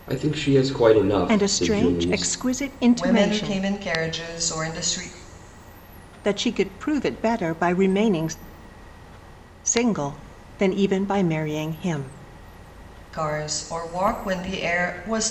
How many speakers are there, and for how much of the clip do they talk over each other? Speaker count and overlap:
3, about 12%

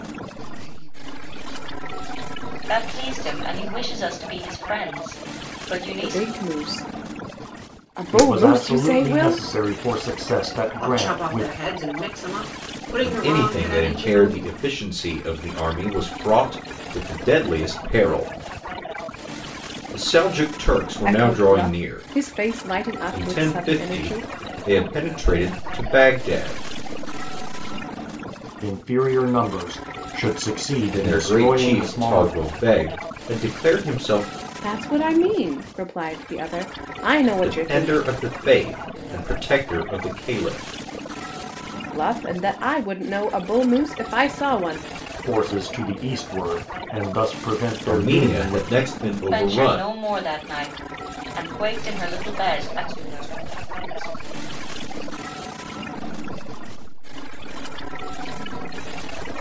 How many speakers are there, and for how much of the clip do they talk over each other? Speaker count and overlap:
6, about 23%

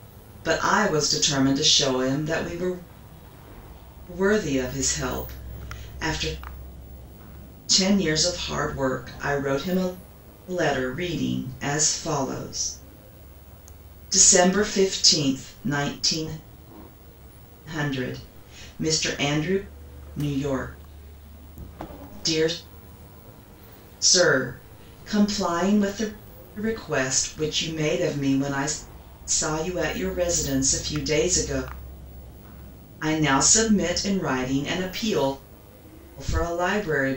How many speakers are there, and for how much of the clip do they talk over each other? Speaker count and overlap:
1, no overlap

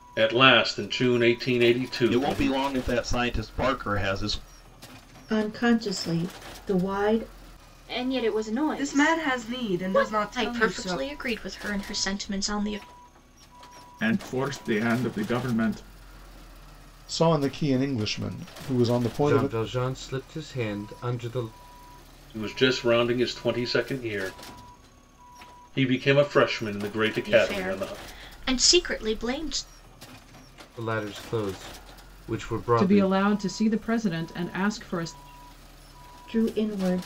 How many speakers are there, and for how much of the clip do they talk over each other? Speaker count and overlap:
9, about 11%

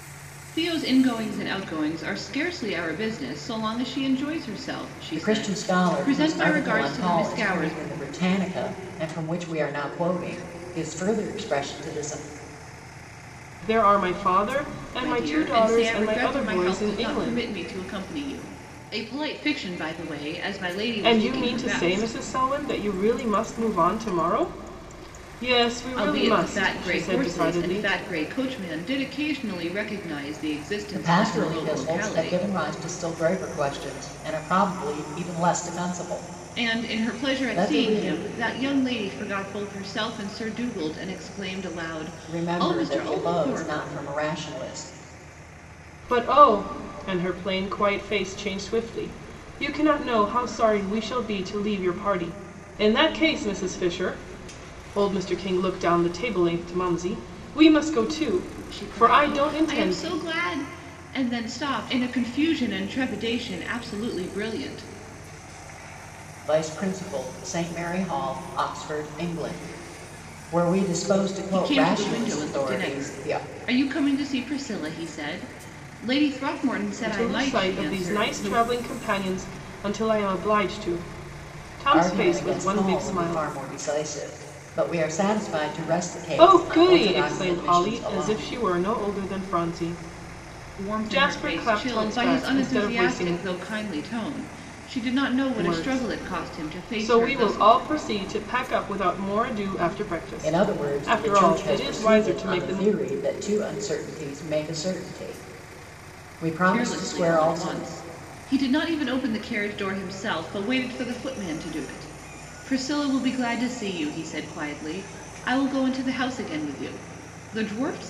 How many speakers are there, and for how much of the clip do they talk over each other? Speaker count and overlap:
3, about 25%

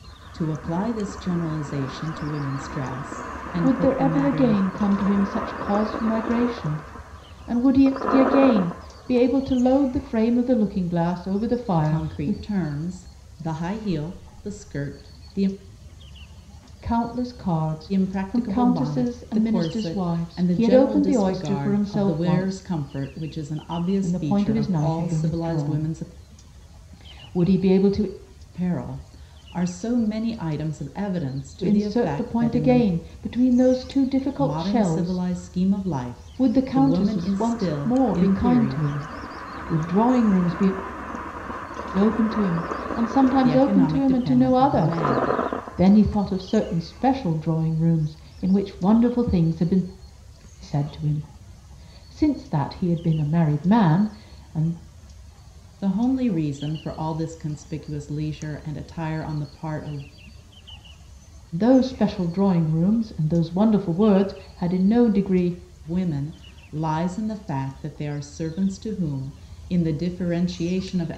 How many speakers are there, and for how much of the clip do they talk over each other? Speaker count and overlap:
2, about 21%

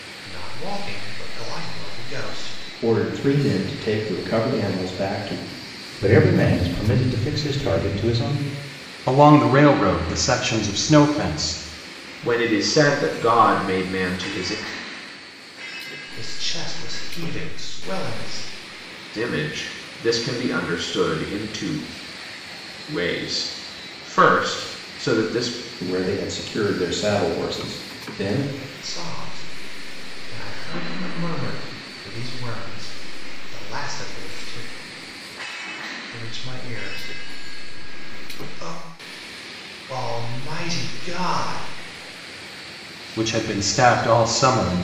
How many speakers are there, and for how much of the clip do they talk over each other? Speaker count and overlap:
5, no overlap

